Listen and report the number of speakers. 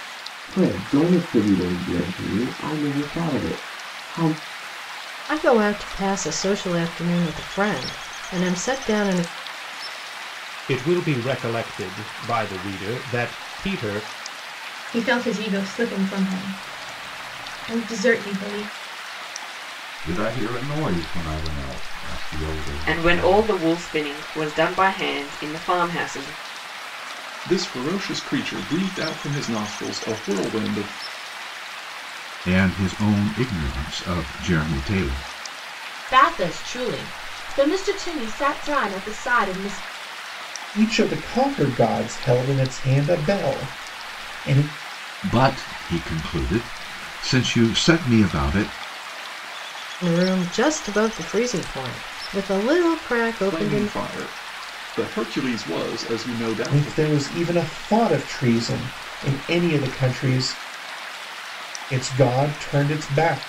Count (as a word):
ten